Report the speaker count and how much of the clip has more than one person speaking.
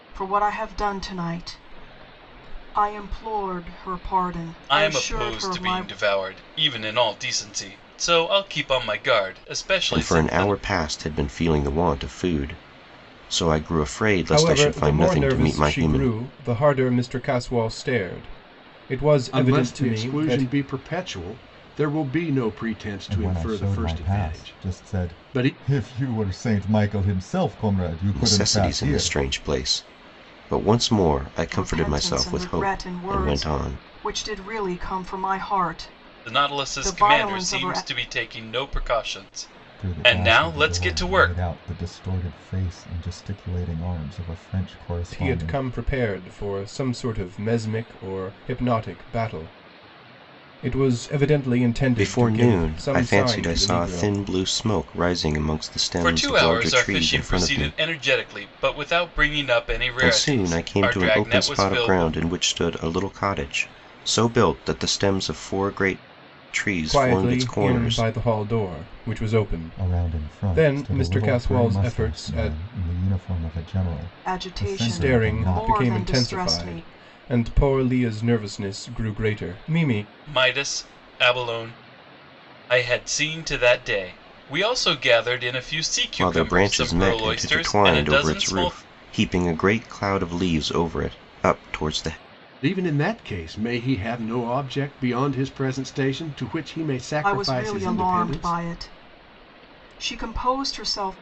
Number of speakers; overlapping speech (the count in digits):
6, about 31%